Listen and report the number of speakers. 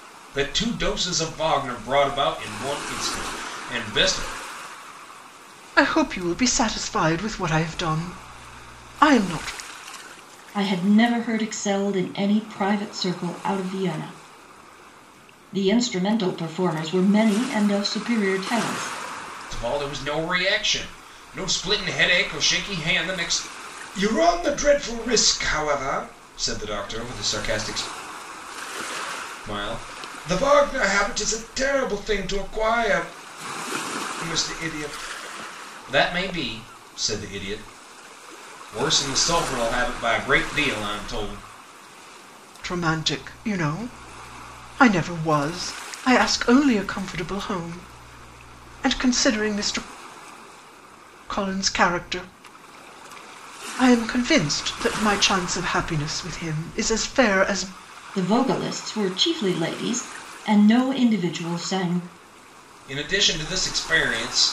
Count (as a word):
three